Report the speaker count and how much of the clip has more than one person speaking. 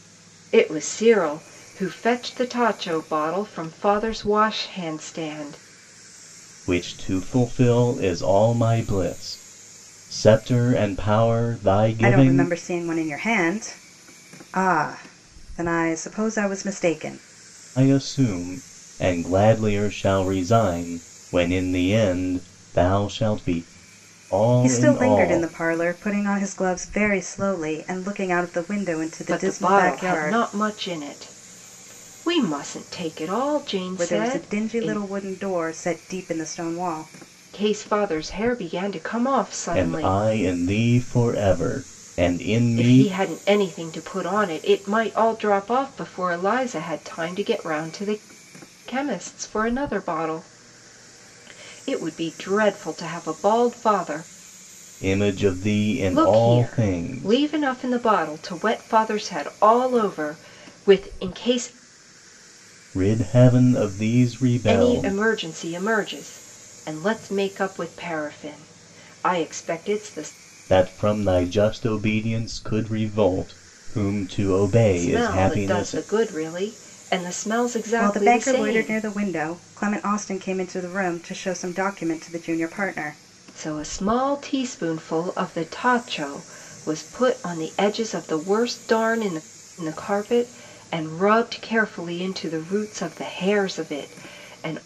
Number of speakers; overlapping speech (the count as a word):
three, about 9%